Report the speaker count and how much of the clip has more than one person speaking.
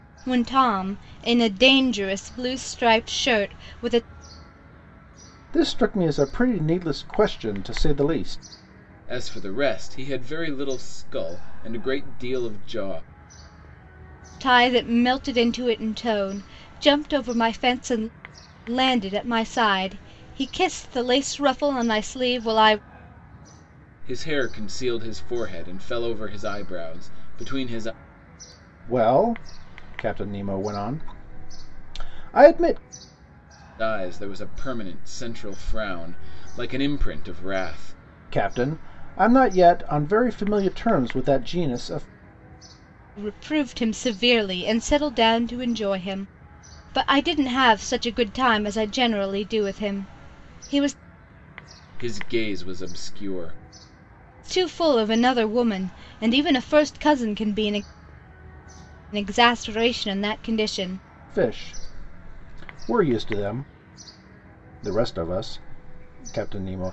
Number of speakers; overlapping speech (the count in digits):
3, no overlap